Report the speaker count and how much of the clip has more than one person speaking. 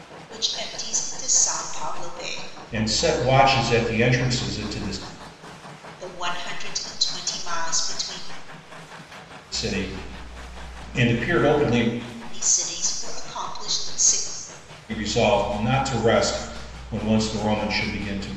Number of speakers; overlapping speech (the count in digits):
2, no overlap